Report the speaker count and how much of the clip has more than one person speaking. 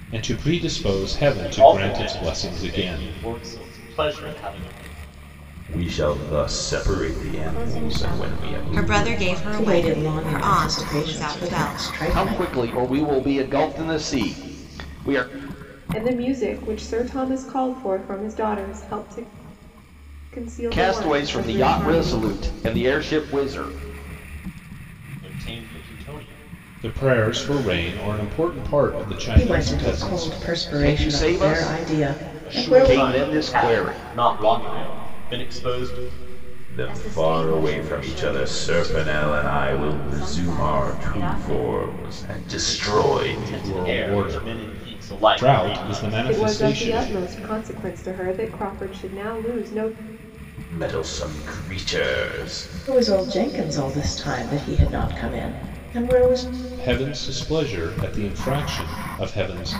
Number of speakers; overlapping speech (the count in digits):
8, about 40%